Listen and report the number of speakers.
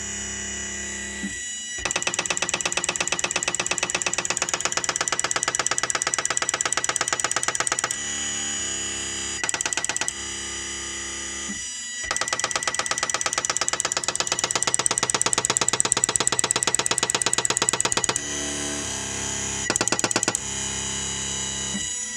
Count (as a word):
zero